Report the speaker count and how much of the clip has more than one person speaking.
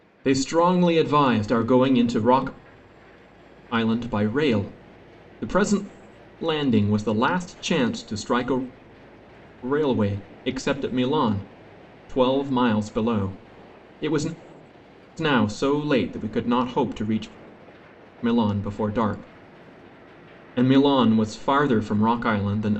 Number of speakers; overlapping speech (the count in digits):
1, no overlap